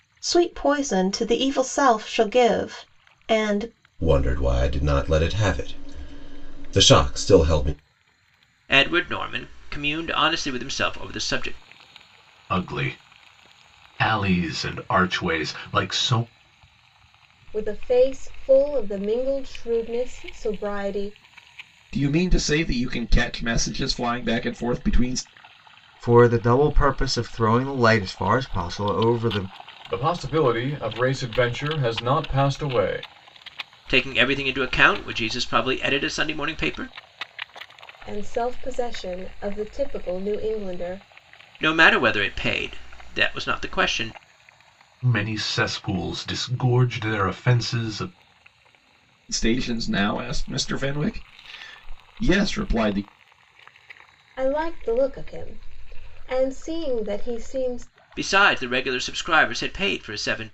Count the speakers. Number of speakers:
eight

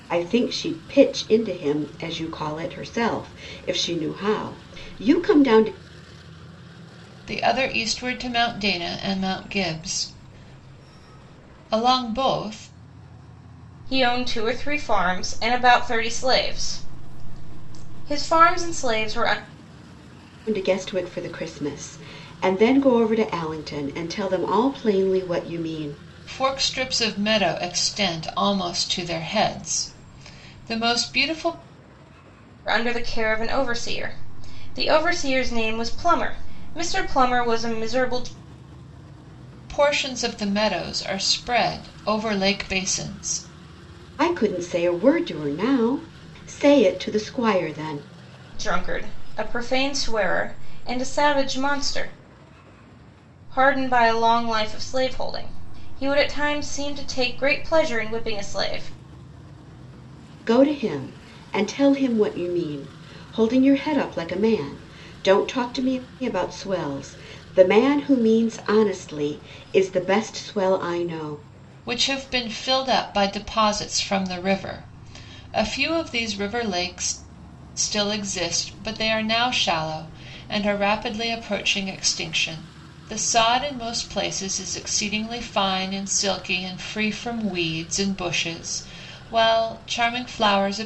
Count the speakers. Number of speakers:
three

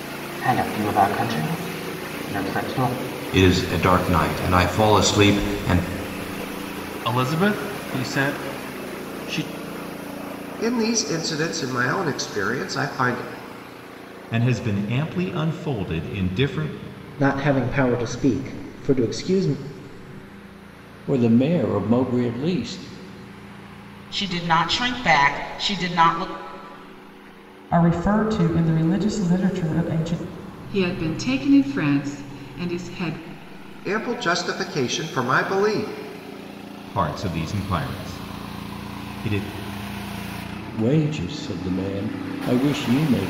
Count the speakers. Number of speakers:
ten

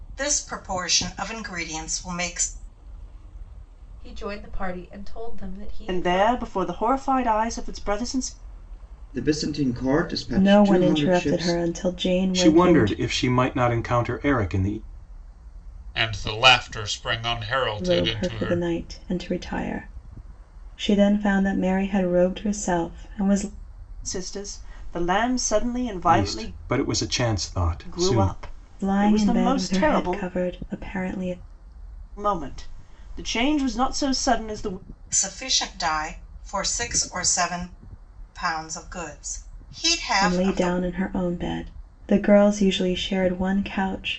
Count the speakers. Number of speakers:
seven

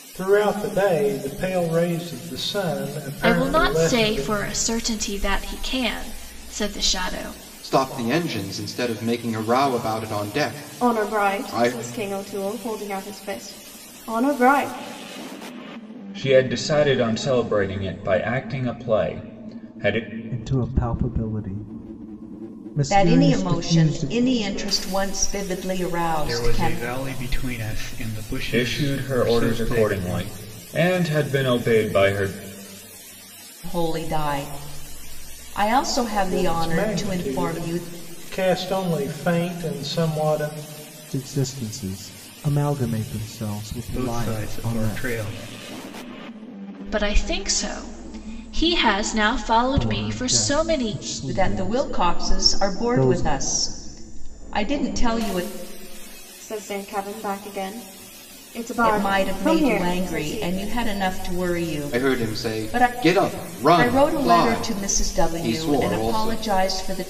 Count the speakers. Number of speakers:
eight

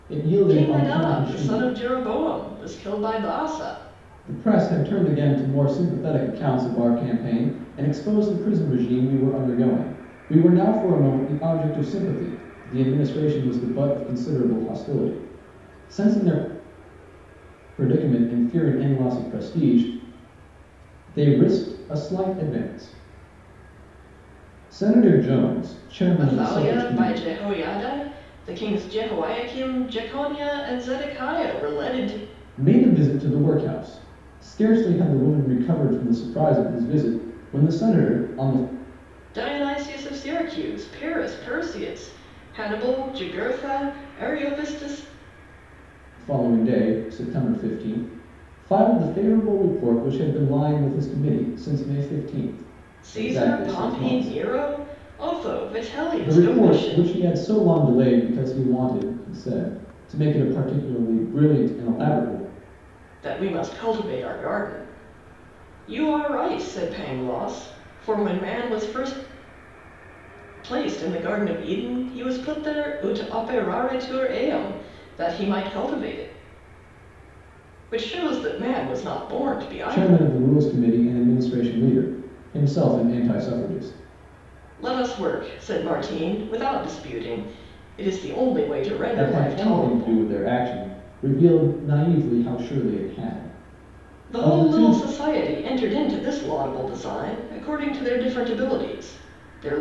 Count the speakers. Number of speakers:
two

